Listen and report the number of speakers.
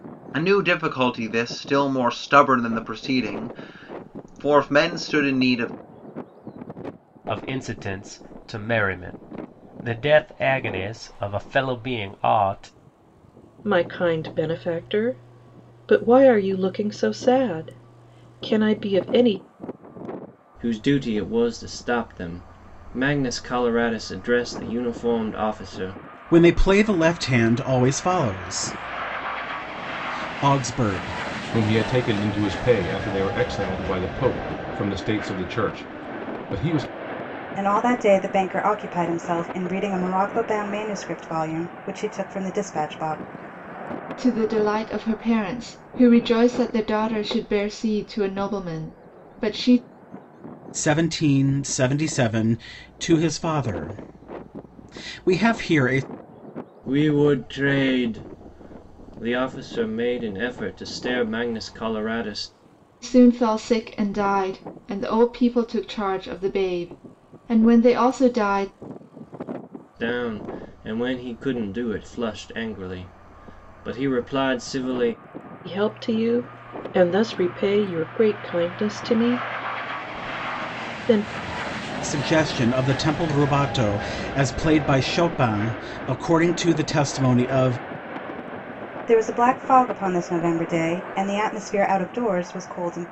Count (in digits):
8